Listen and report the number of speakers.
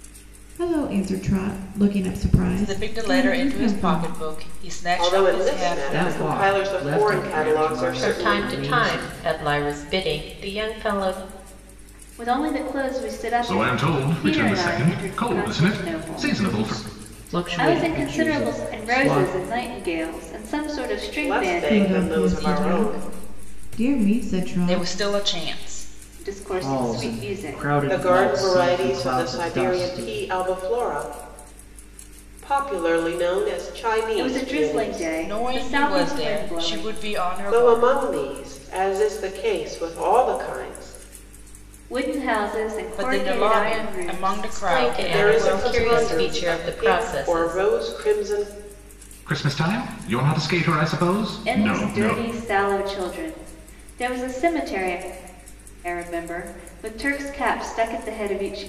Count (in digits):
7